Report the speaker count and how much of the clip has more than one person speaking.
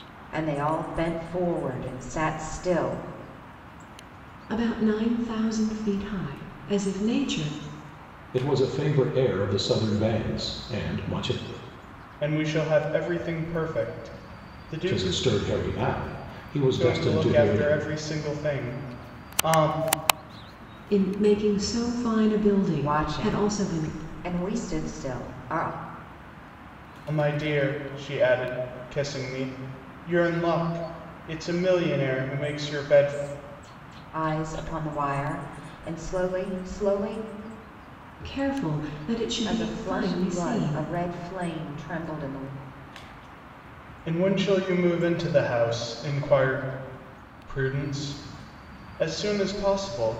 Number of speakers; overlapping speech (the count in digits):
4, about 8%